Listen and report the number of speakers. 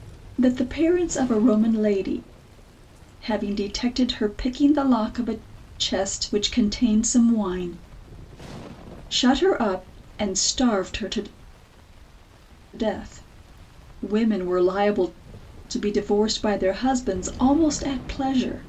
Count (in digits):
1